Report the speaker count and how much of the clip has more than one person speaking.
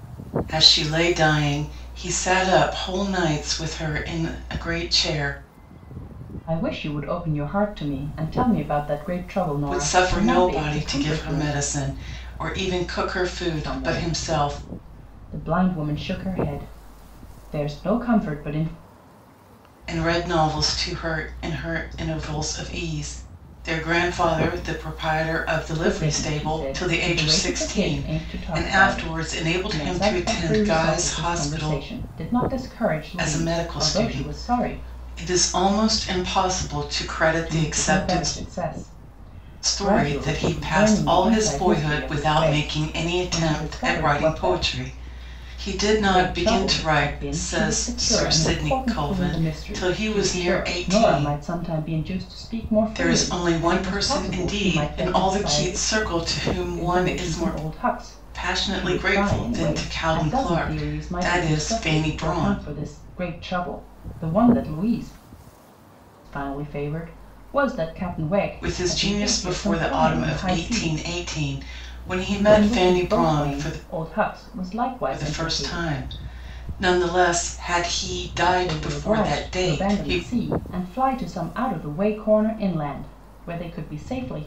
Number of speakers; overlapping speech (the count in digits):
2, about 42%